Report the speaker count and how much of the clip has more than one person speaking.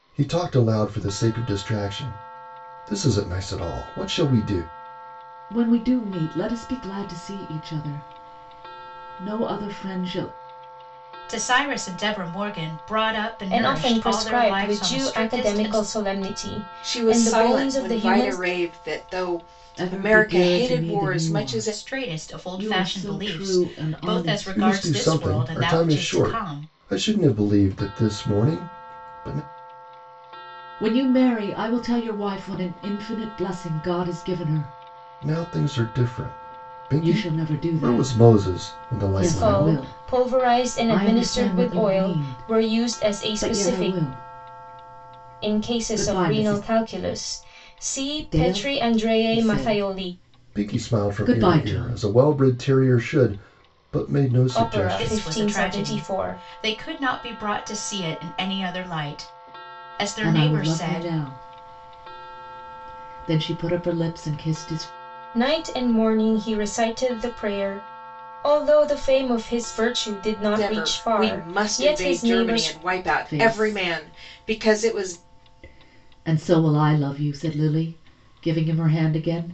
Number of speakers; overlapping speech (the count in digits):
5, about 37%